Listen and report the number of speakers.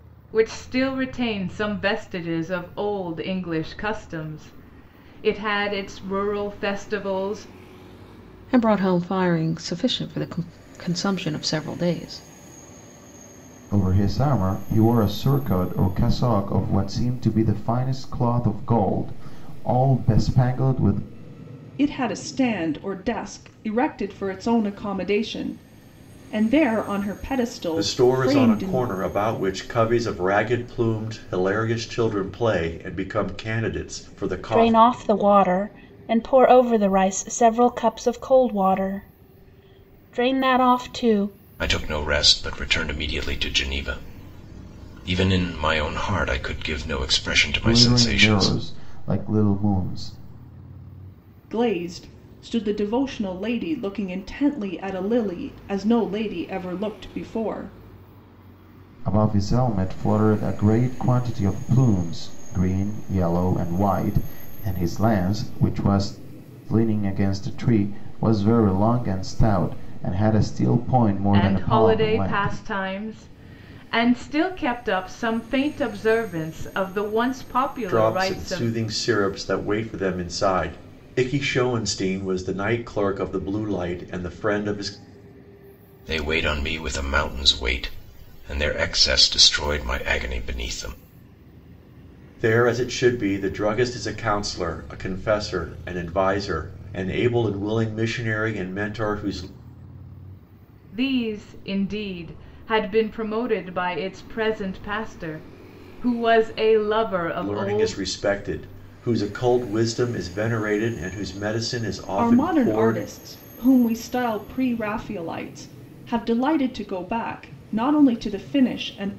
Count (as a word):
seven